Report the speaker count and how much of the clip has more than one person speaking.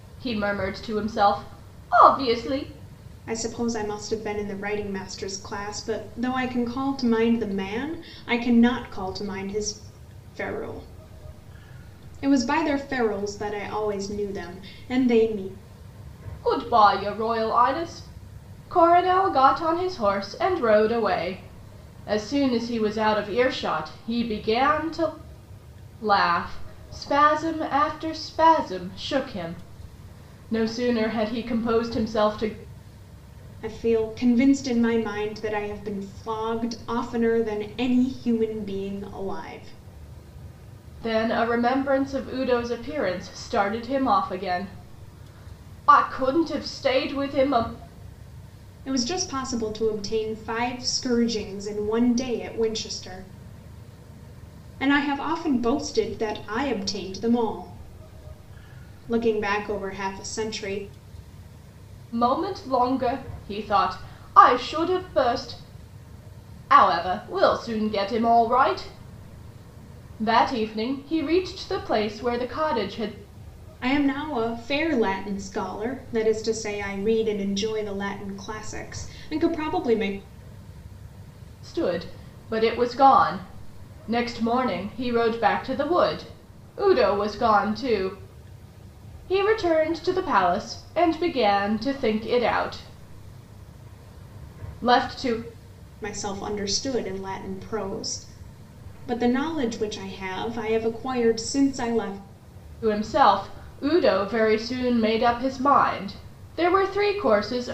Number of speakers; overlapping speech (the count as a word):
two, no overlap